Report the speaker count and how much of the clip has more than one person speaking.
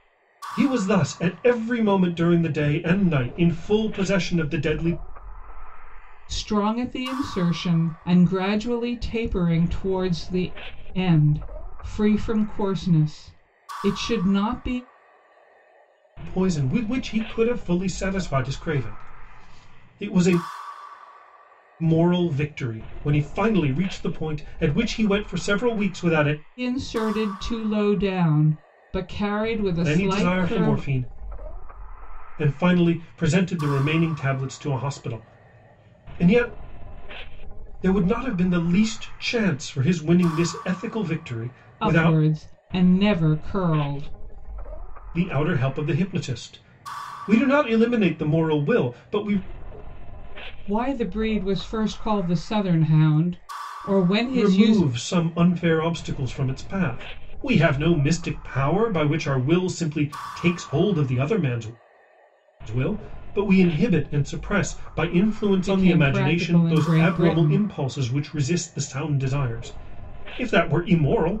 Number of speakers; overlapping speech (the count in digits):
2, about 6%